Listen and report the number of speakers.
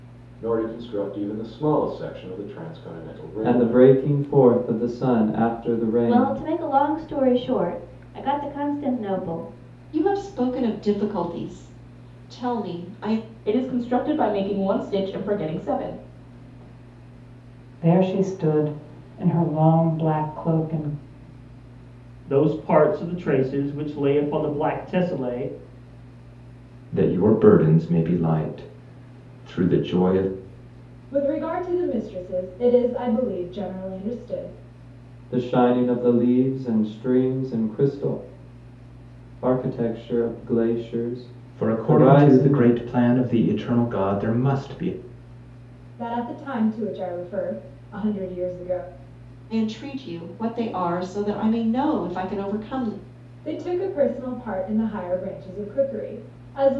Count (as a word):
nine